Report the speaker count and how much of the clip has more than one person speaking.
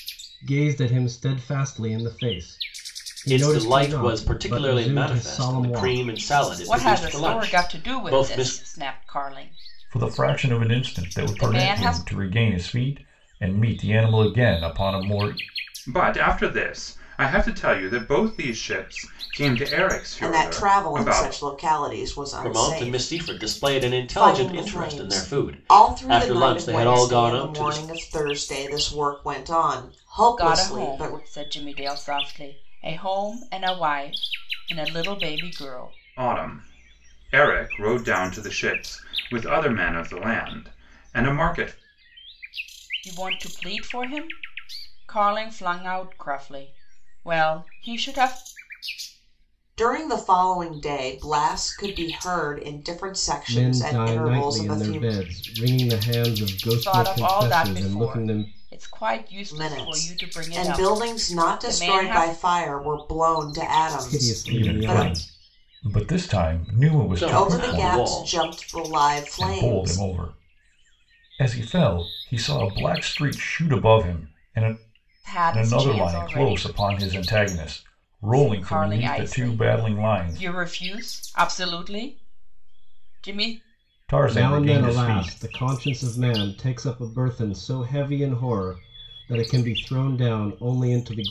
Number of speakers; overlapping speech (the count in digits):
6, about 31%